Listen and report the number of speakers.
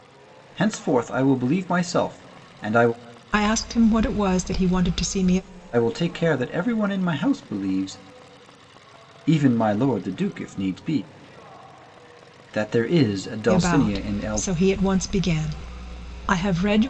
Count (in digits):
2